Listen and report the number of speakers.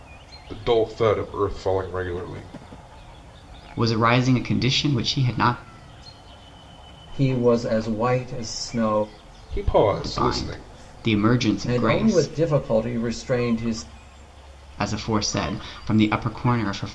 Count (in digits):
3